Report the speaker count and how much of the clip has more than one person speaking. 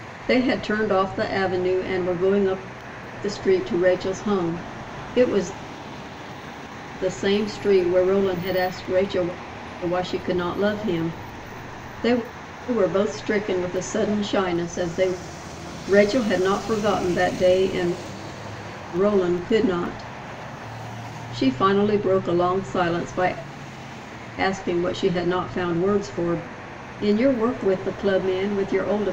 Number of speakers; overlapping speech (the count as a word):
one, no overlap